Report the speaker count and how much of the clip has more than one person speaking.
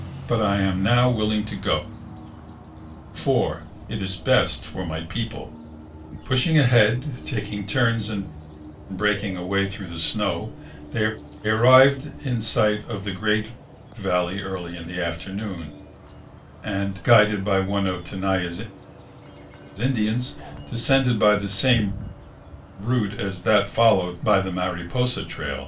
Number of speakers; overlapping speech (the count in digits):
1, no overlap